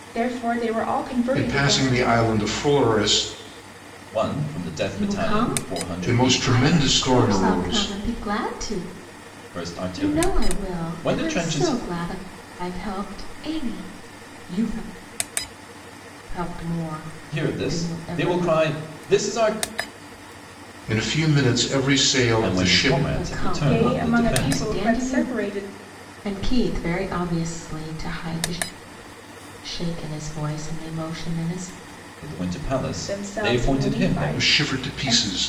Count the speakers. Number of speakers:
four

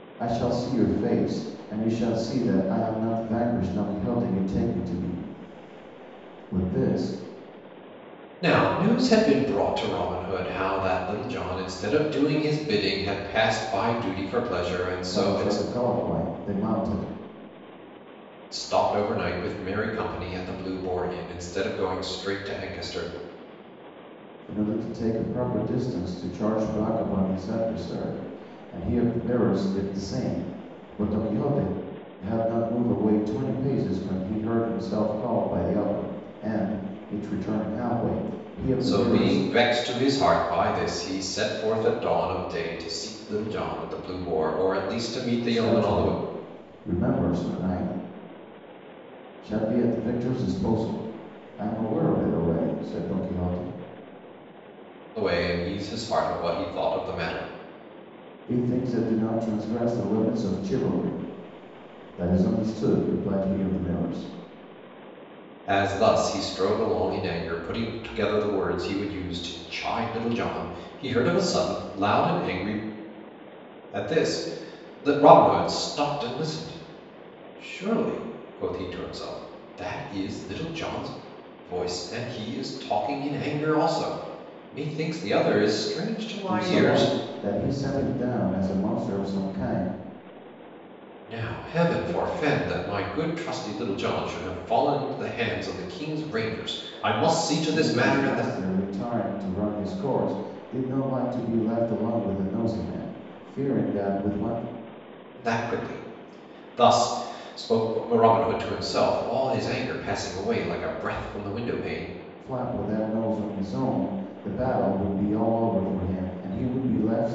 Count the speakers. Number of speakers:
two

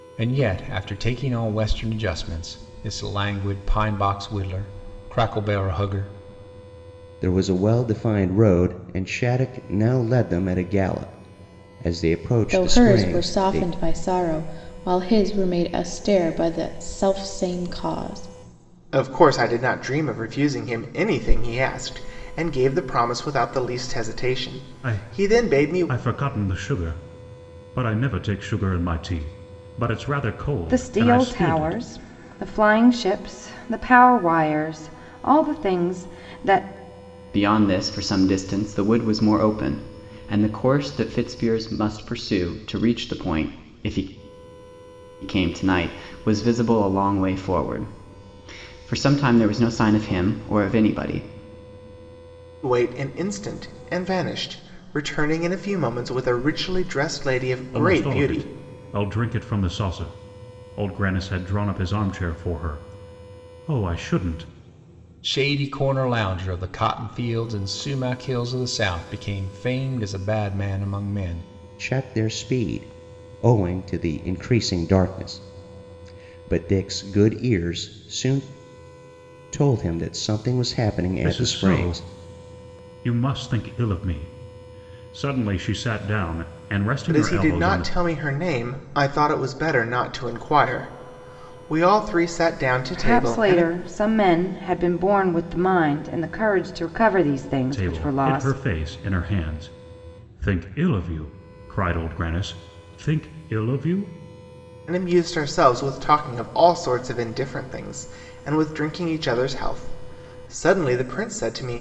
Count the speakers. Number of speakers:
seven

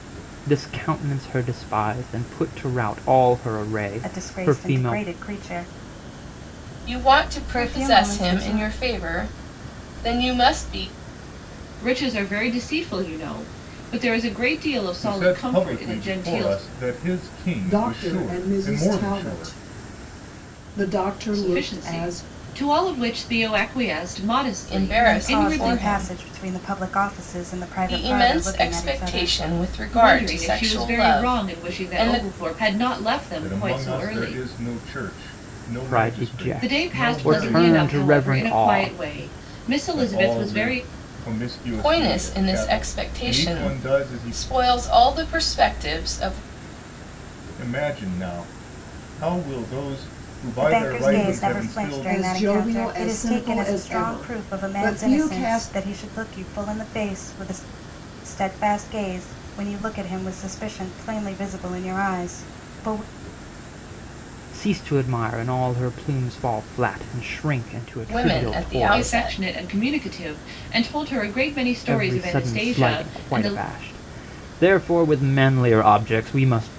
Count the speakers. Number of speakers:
six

